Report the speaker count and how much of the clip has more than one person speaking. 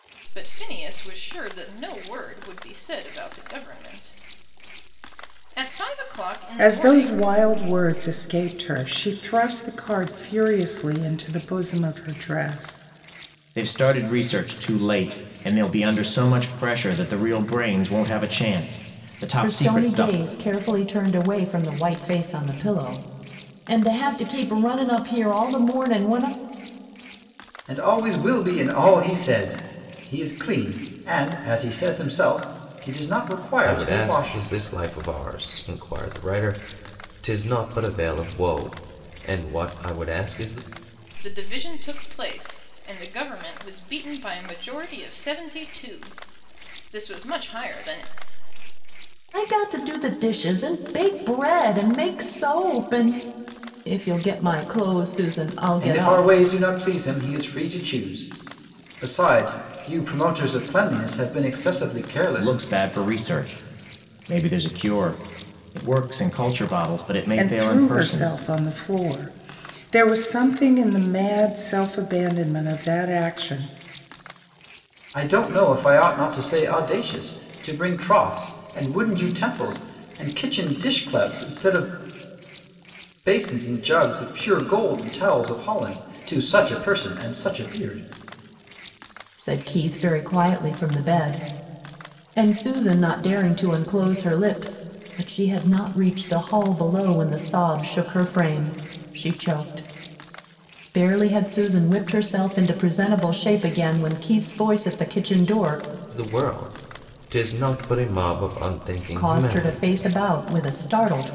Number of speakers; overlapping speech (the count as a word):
six, about 4%